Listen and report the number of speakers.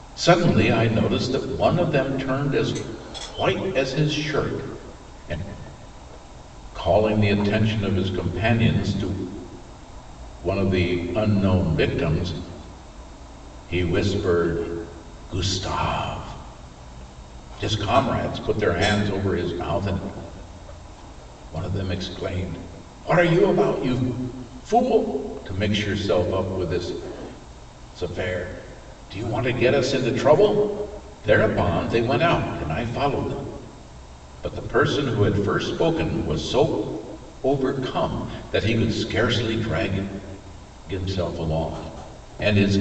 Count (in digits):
1